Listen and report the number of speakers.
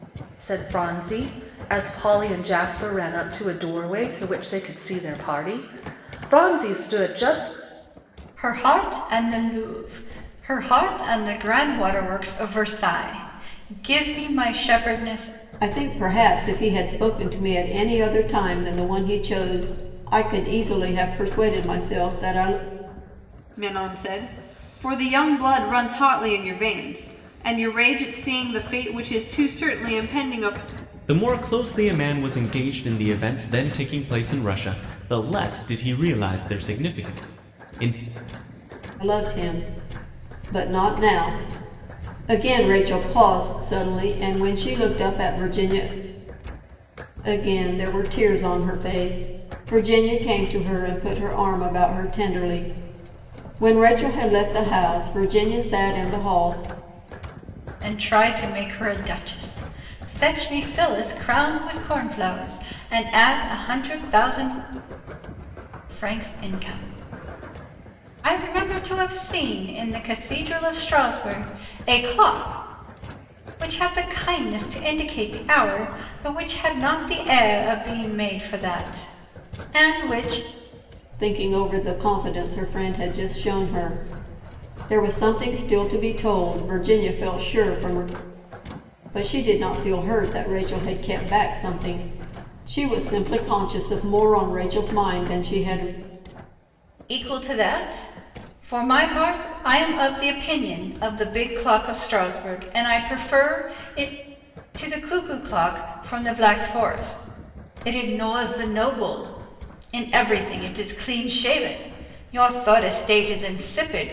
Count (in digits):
5